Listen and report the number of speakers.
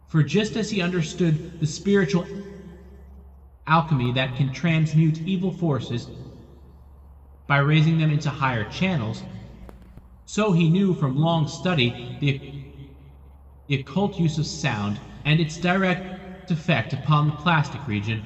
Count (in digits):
1